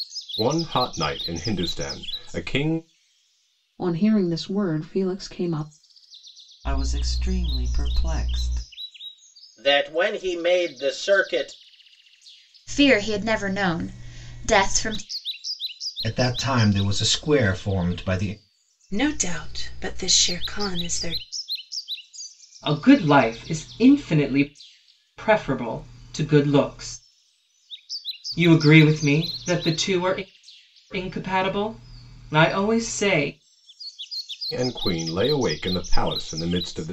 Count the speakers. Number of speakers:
8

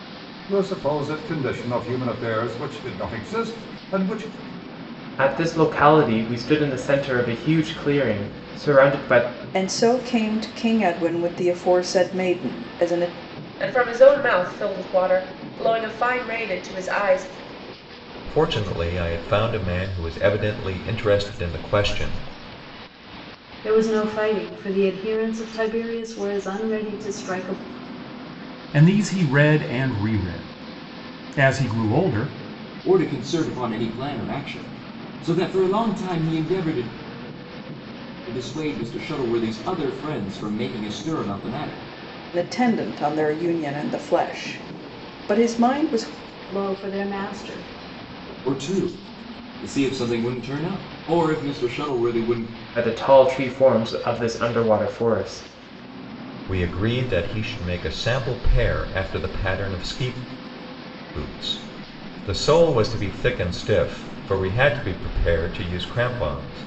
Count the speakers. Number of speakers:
8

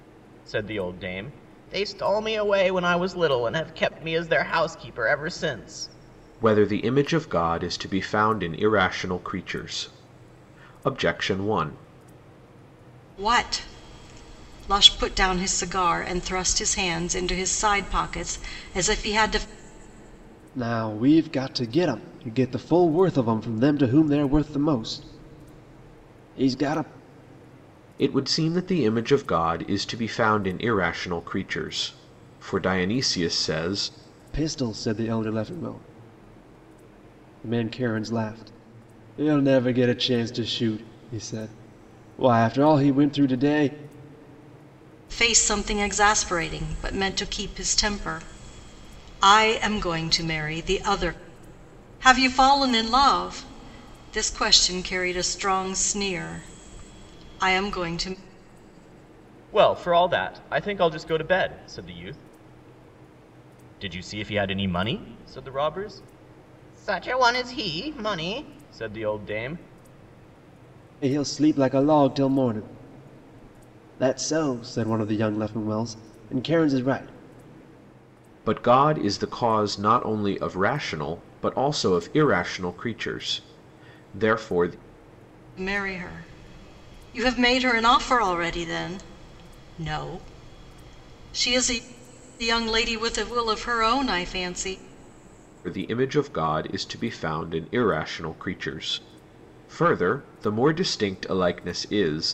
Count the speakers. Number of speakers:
4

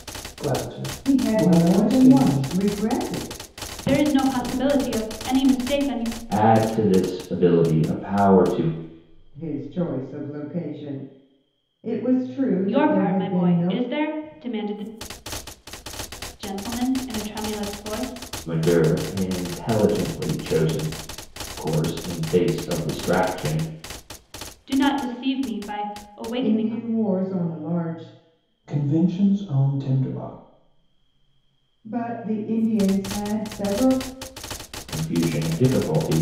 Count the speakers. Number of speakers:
4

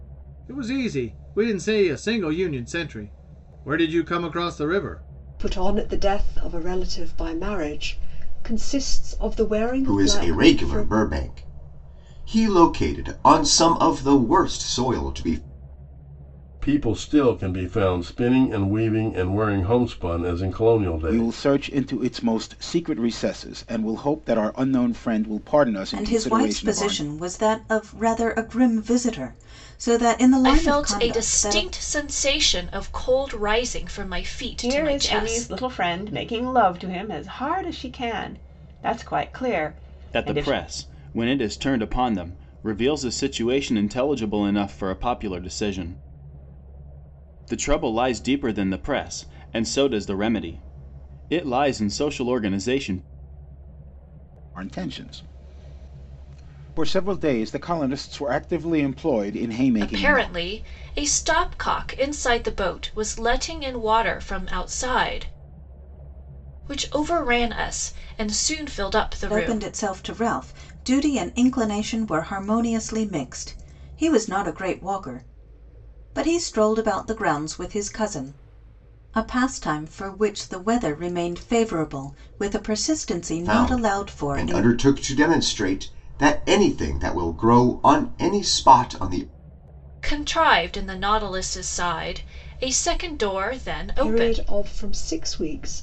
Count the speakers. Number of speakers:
9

